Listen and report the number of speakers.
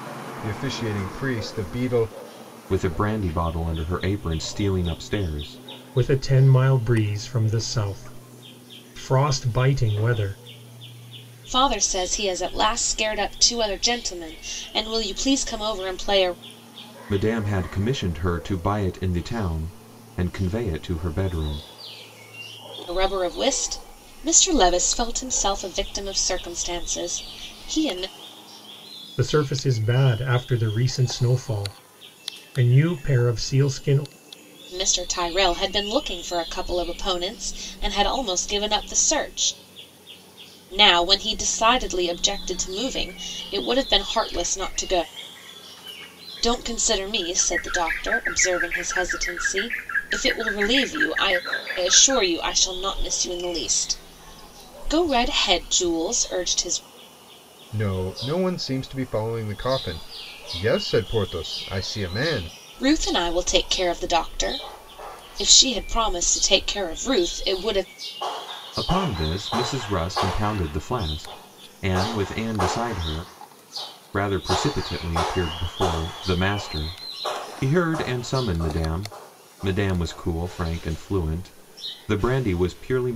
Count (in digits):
4